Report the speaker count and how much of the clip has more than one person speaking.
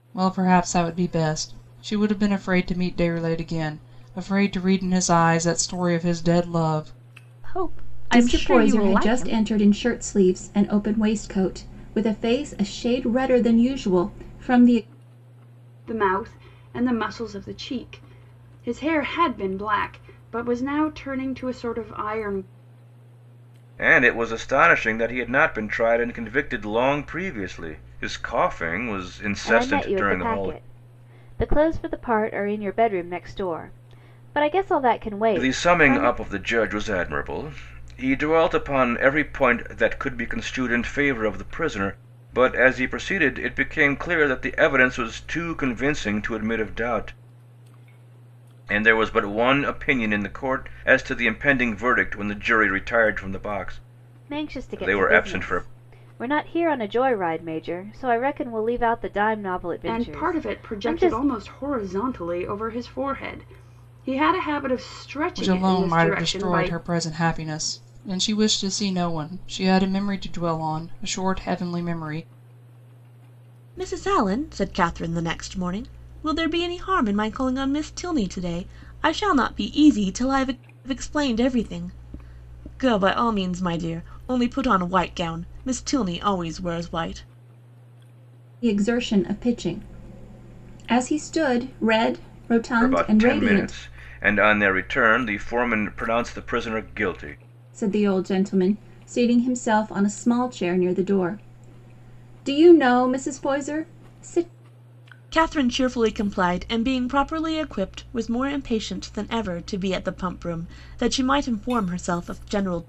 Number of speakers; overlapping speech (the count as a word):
six, about 8%